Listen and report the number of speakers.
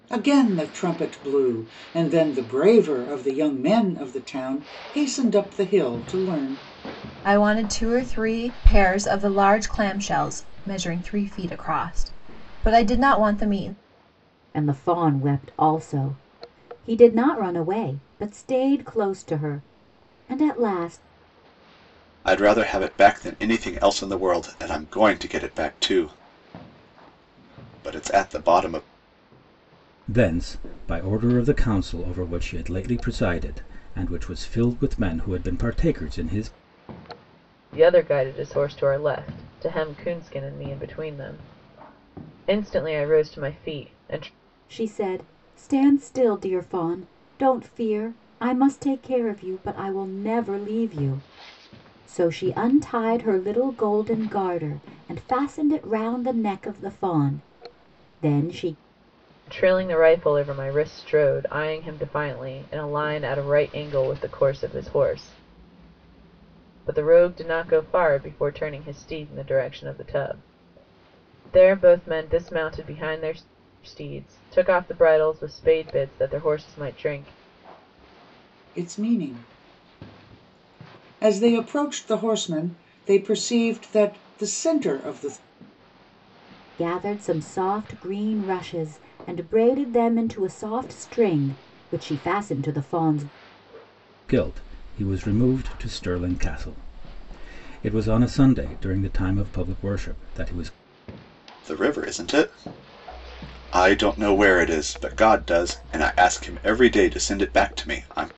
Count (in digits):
6